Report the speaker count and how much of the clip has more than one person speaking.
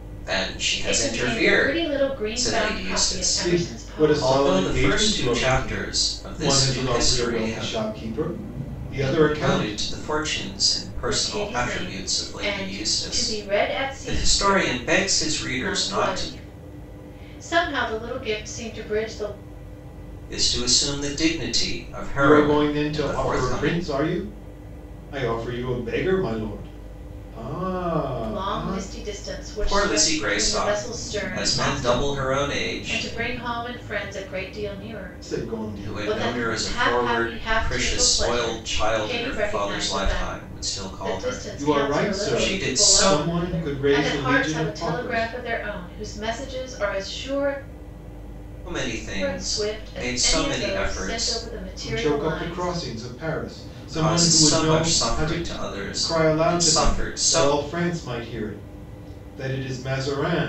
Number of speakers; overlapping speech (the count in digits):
3, about 55%